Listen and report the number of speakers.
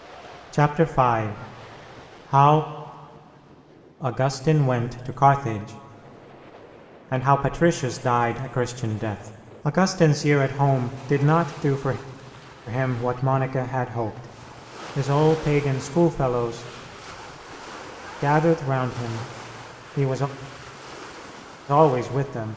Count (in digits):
1